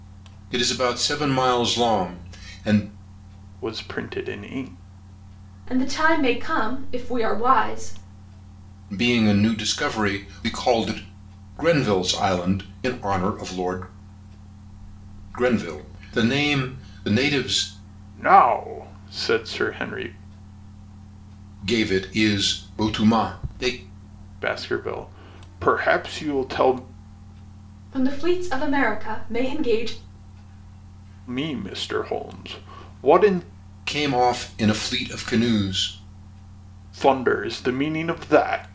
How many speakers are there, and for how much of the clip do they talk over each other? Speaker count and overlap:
3, no overlap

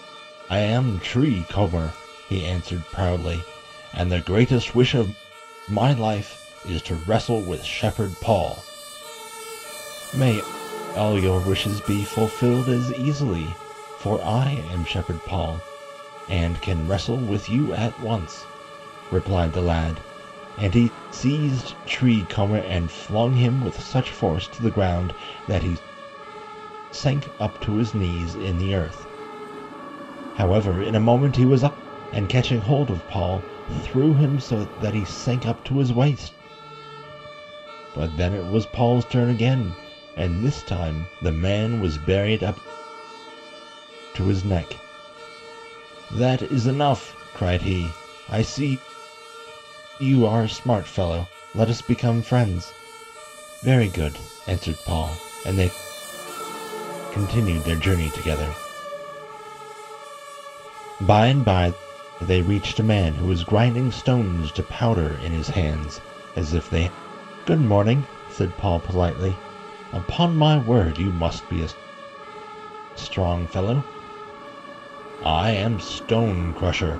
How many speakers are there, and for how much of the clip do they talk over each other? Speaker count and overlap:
1, no overlap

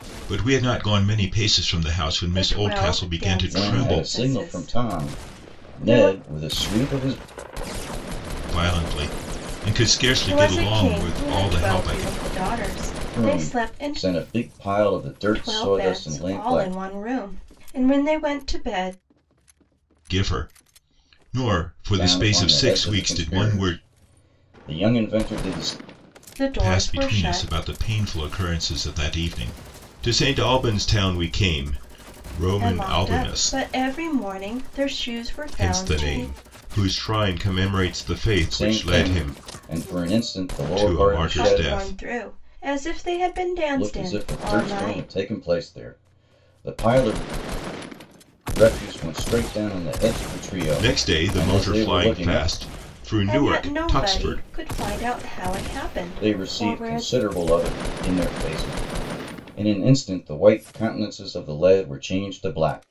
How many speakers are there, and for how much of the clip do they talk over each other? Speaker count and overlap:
3, about 32%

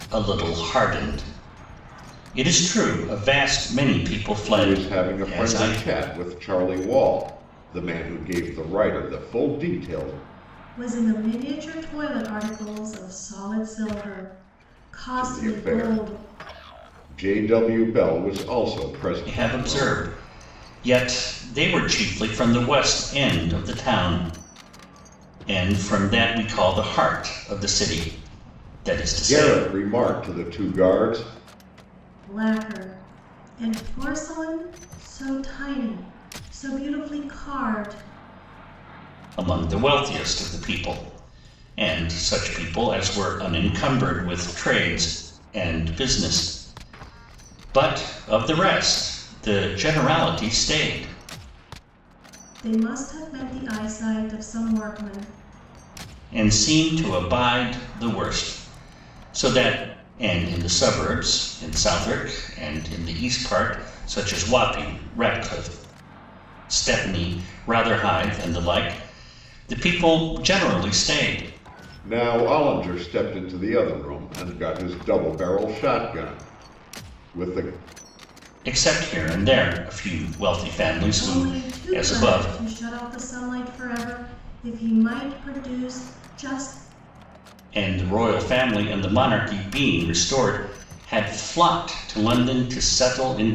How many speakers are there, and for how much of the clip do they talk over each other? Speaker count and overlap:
3, about 5%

